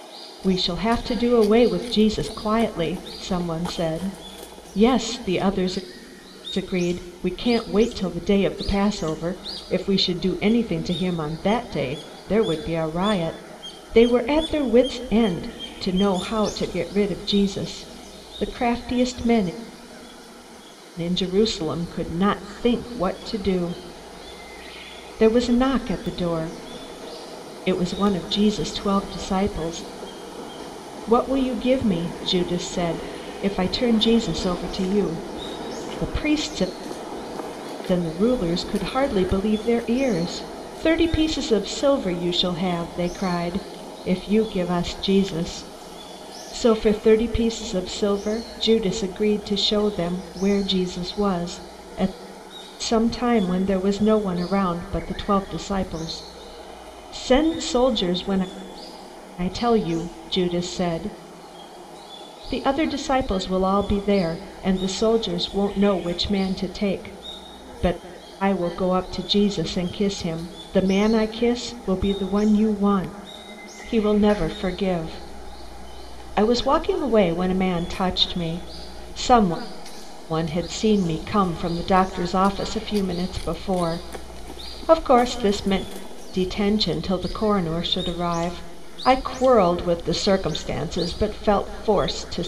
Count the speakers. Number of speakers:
one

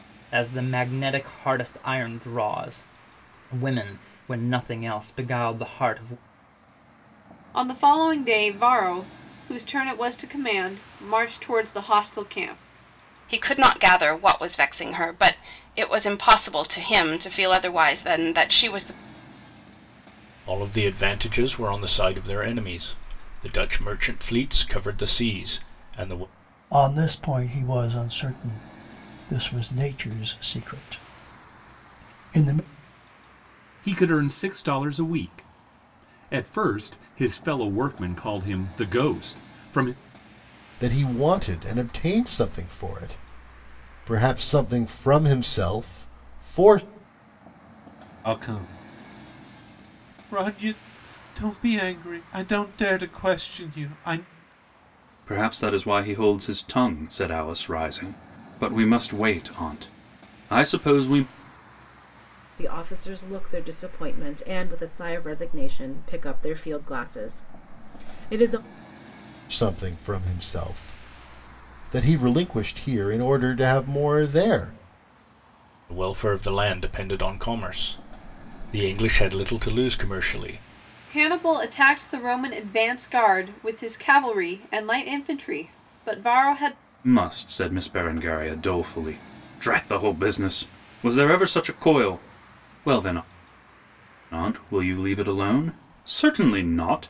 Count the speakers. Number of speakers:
ten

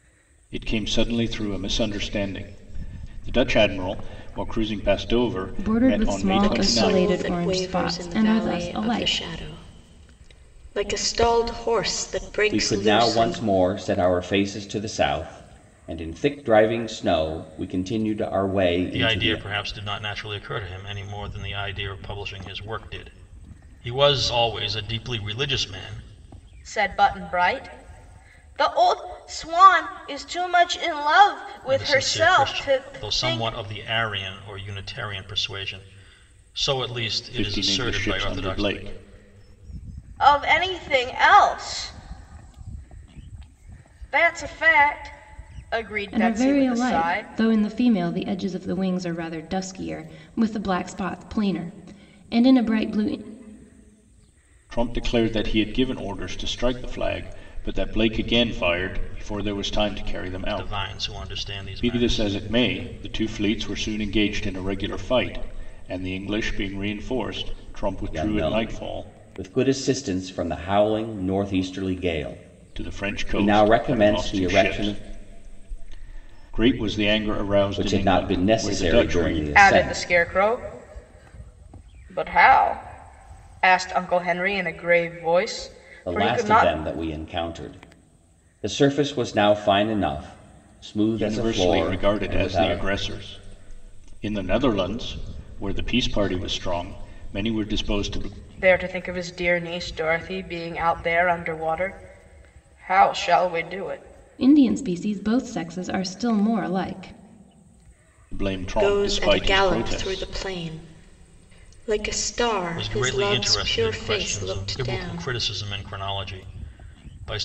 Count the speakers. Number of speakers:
six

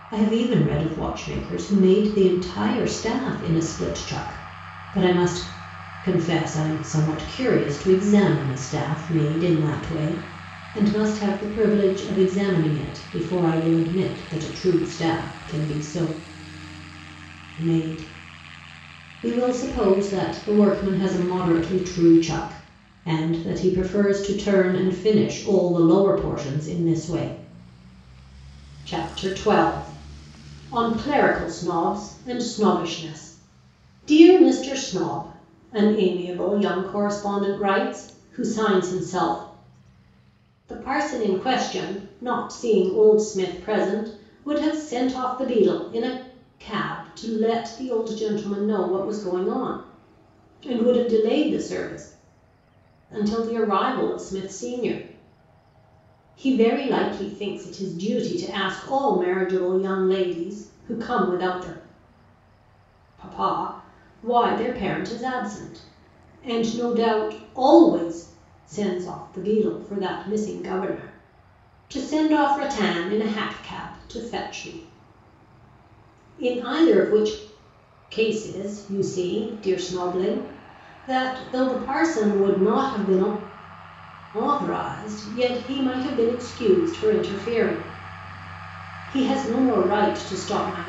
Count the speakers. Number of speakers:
one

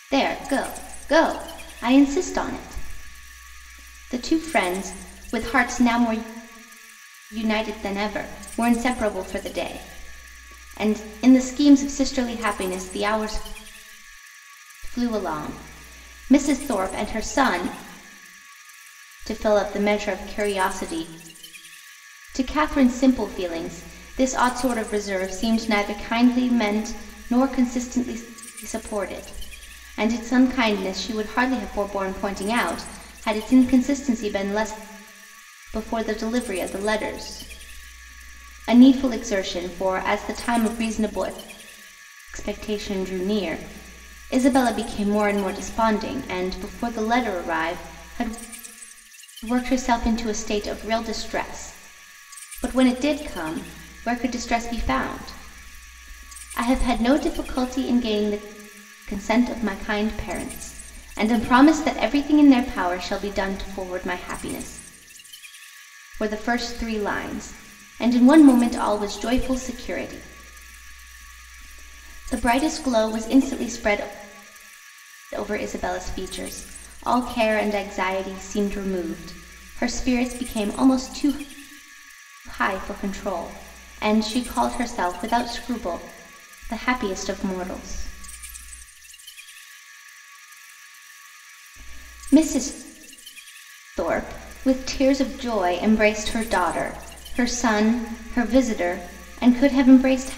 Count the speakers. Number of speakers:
one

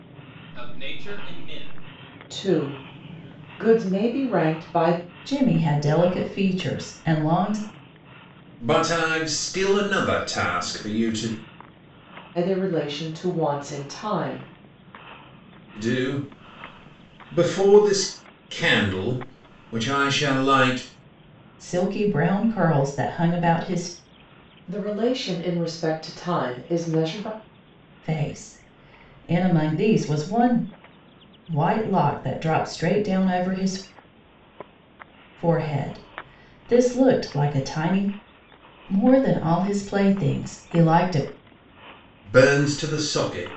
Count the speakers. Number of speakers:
four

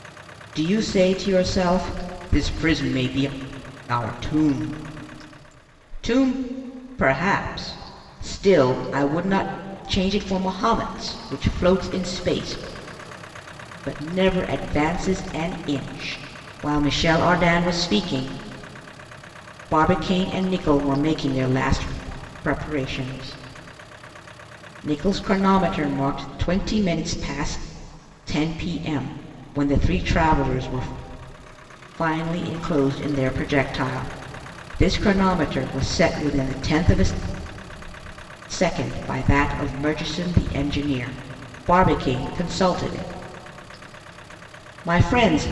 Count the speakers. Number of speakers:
one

